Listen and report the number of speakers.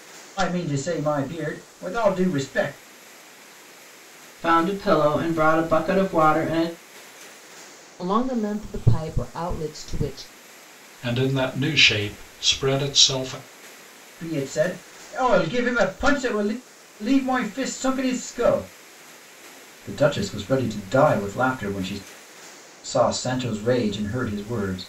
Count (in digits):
4